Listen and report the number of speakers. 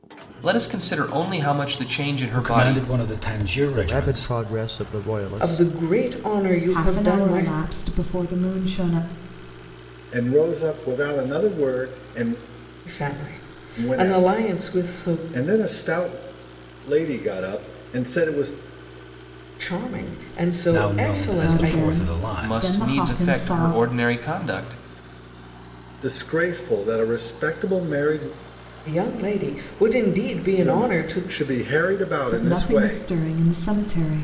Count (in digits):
6